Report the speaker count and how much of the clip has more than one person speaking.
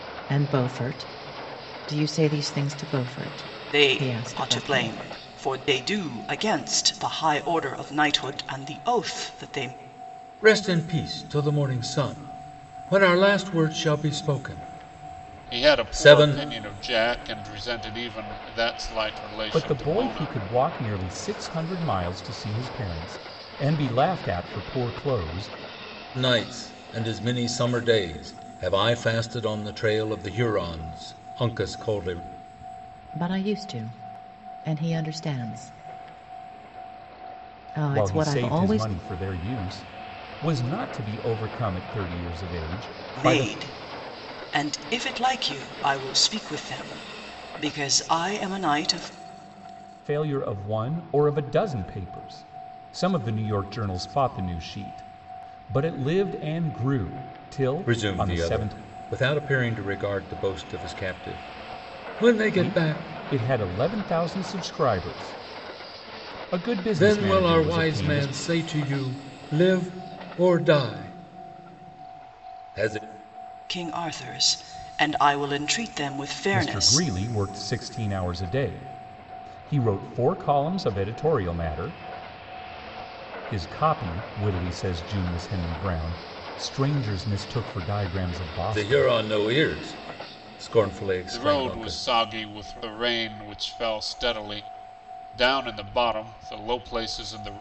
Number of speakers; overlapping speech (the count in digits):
5, about 10%